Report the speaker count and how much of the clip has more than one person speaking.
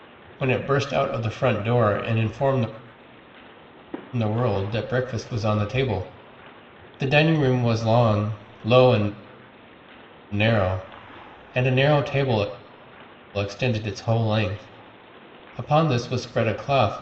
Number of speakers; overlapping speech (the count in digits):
1, no overlap